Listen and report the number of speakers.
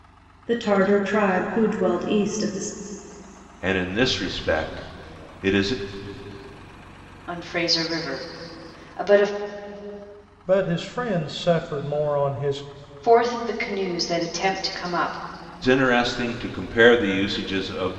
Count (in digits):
4